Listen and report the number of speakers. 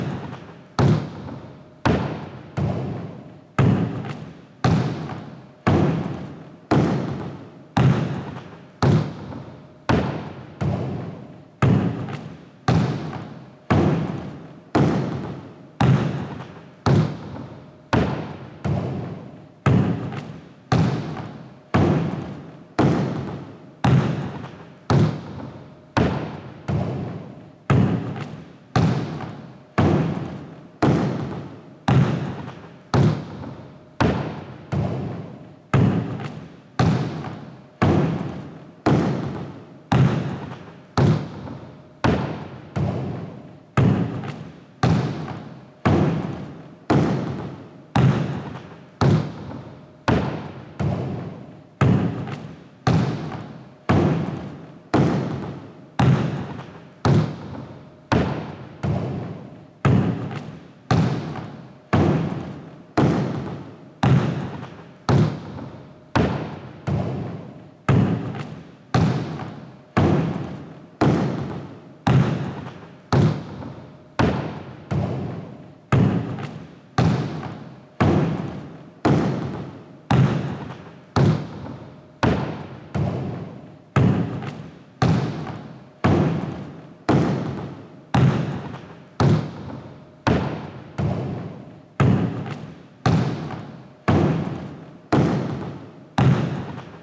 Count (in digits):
0